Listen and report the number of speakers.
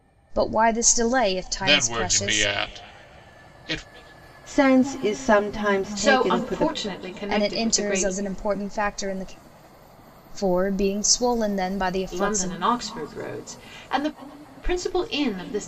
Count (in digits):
4